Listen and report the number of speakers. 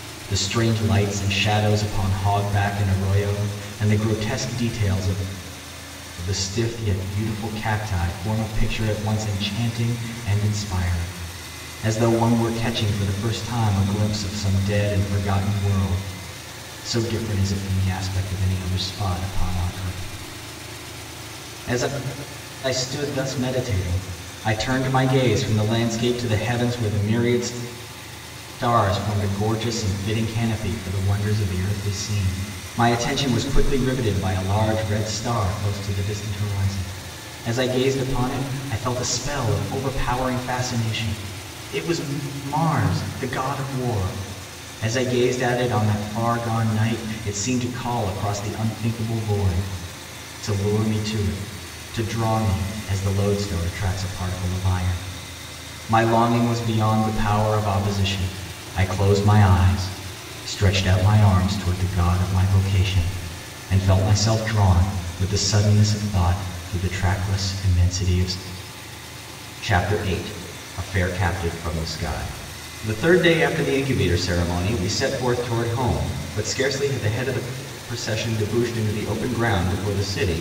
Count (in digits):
1